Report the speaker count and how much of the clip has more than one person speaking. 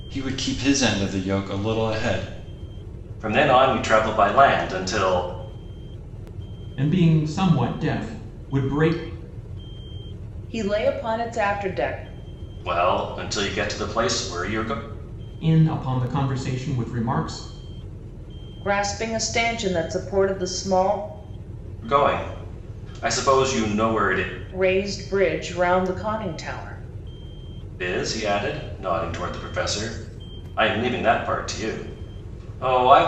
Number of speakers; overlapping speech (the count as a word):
four, no overlap